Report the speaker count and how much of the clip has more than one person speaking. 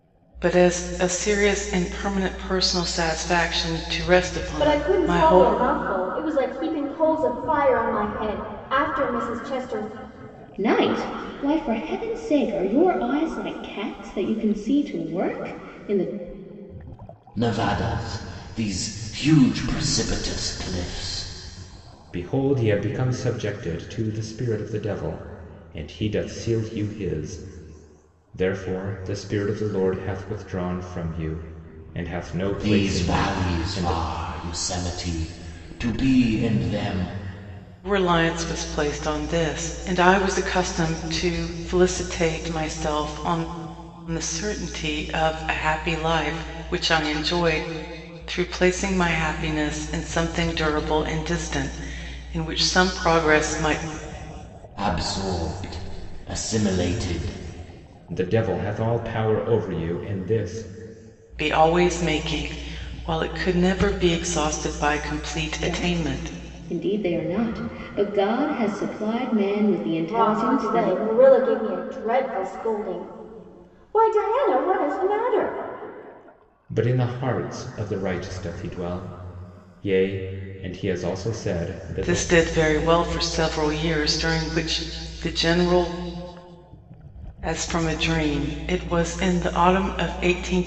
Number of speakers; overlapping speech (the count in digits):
5, about 5%